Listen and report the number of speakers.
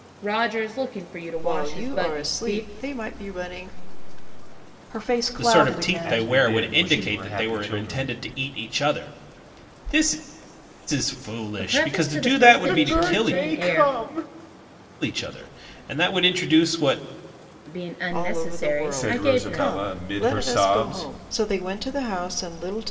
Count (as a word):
five